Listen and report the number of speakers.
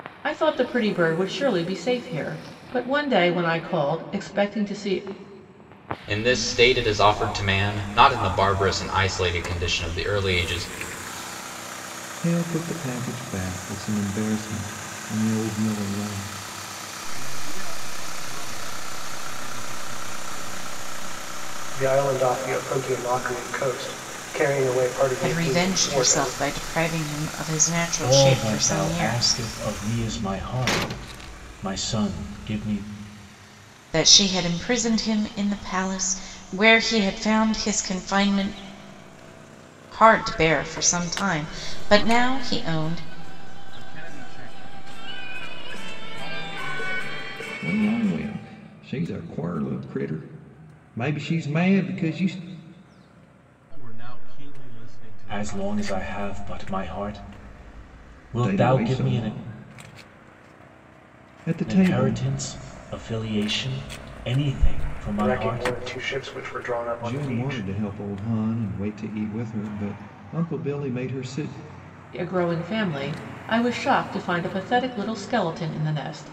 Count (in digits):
7